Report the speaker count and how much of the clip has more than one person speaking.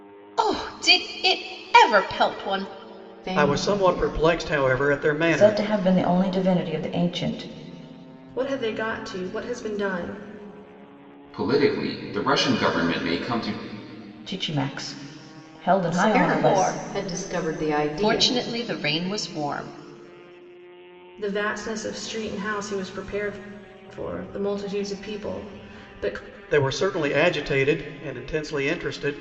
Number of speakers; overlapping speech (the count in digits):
6, about 8%